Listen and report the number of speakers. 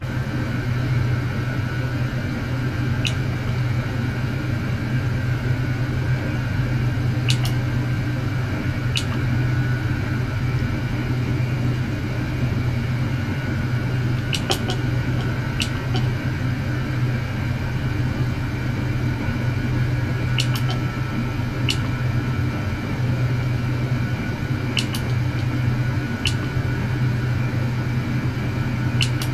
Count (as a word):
zero